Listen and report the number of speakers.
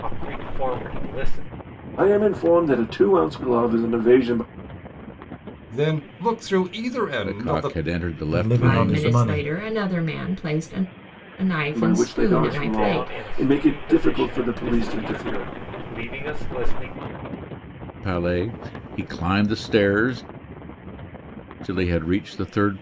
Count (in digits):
6